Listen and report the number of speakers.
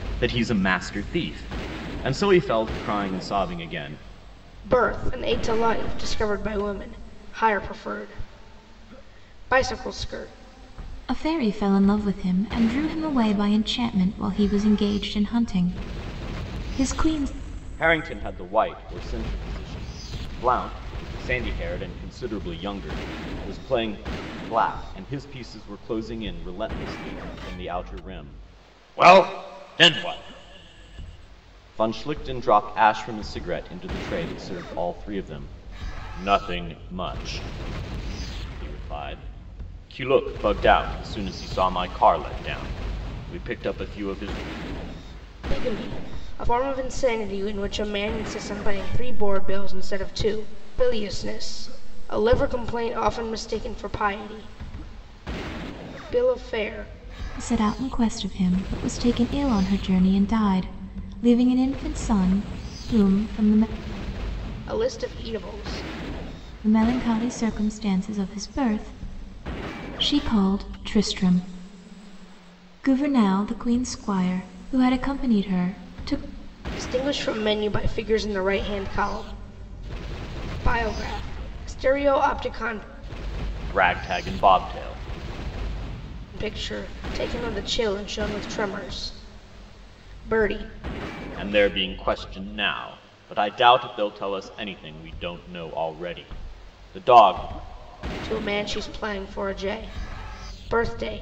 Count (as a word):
three